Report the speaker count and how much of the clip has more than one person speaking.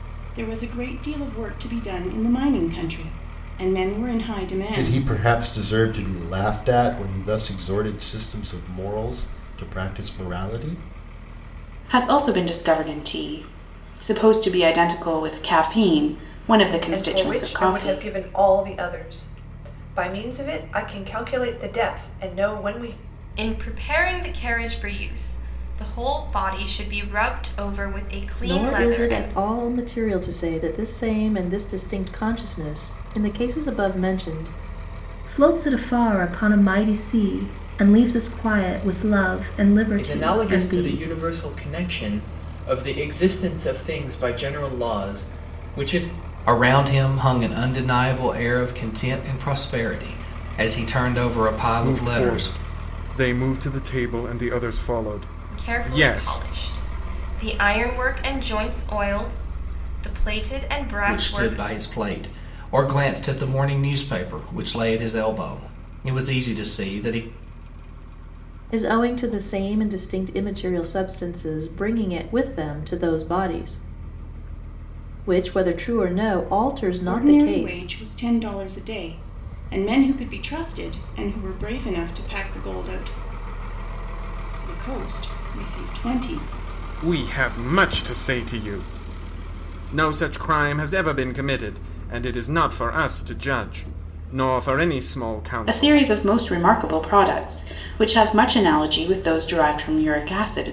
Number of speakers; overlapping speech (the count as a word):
ten, about 8%